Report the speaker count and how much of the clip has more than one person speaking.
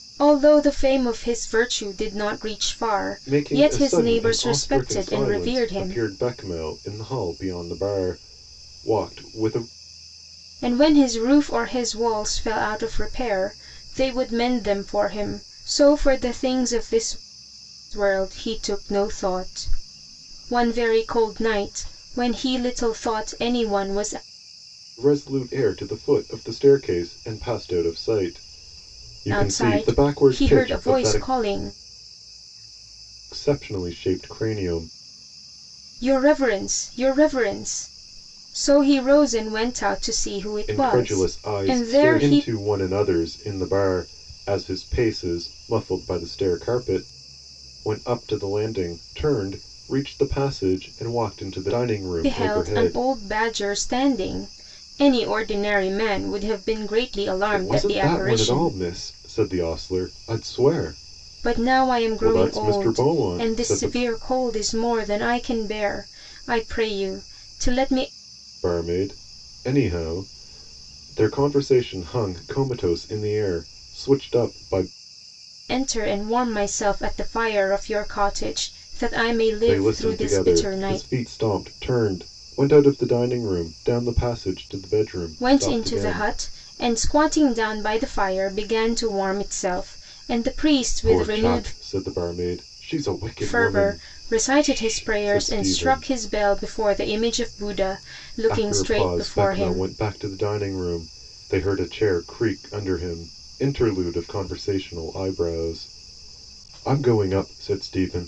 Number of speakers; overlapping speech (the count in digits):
2, about 17%